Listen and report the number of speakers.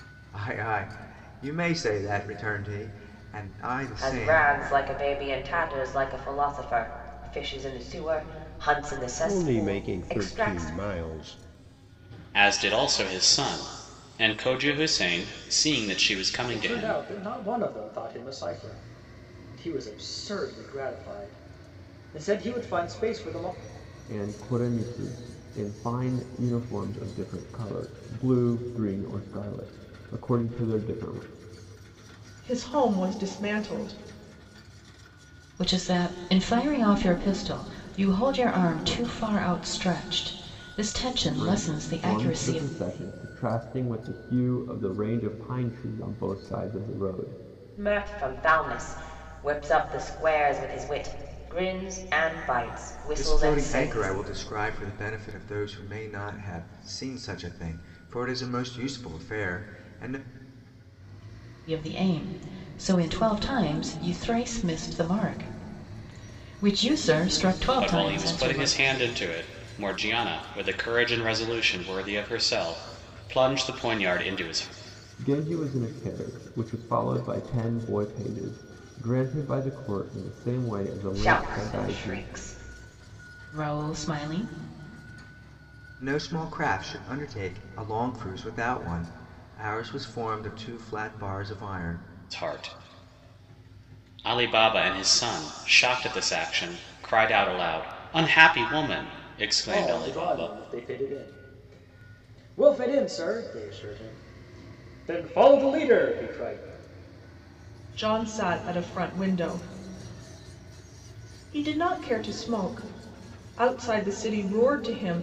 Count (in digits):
8